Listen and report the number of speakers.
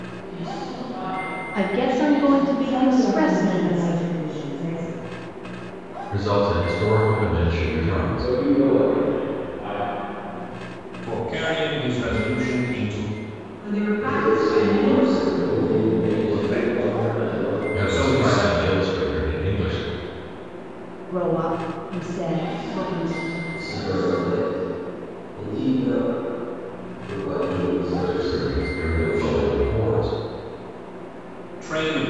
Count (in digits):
8